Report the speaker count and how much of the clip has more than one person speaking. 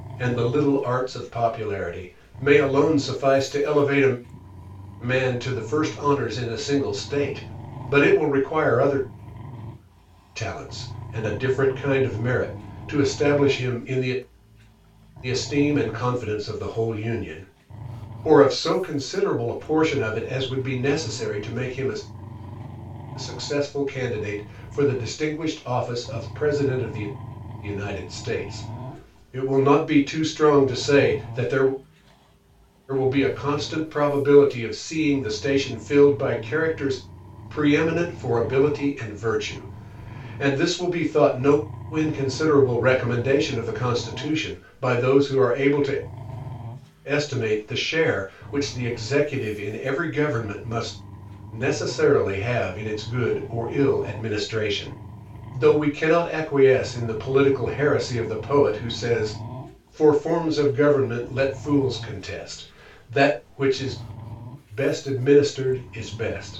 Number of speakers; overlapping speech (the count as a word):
one, no overlap